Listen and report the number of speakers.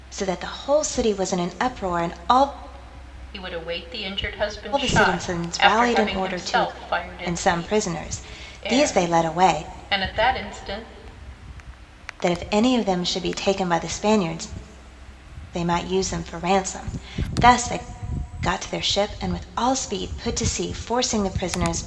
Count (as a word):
two